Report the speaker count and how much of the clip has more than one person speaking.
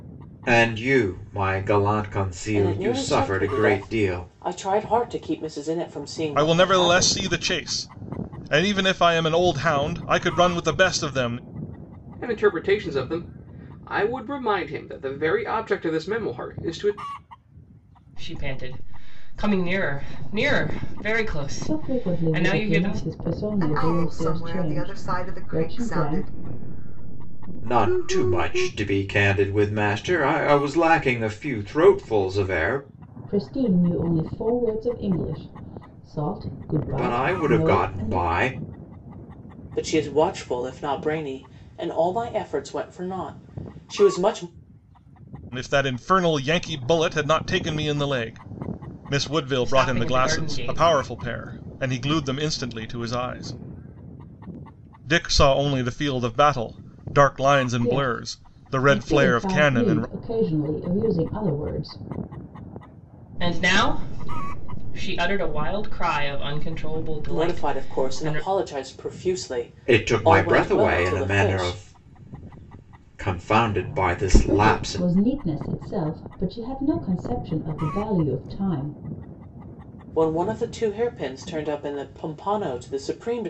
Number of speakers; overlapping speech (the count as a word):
seven, about 20%